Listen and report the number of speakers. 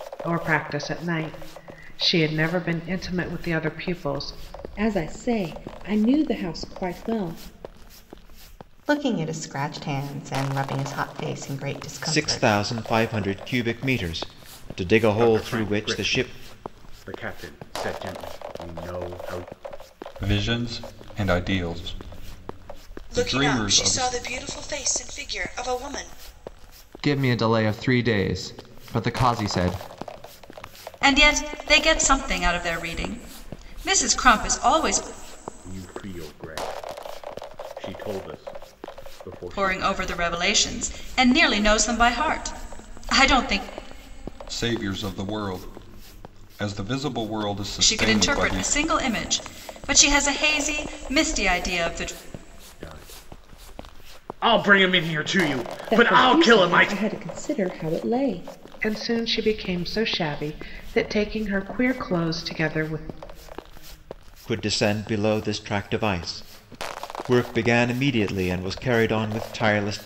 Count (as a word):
nine